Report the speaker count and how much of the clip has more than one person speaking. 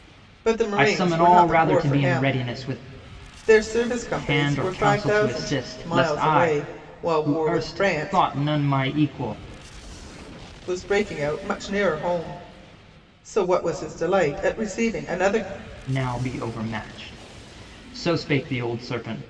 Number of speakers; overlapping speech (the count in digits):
2, about 25%